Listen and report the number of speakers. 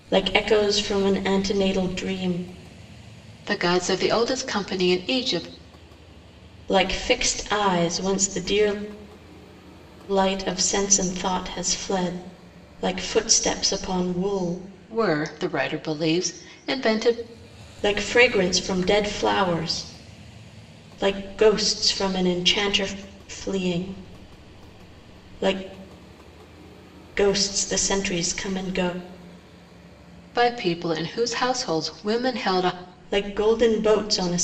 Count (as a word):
two